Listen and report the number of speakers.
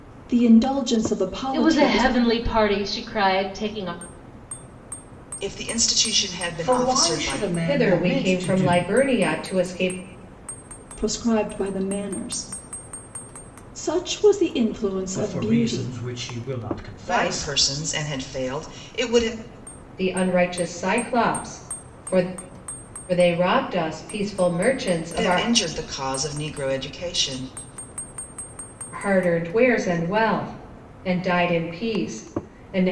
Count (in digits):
5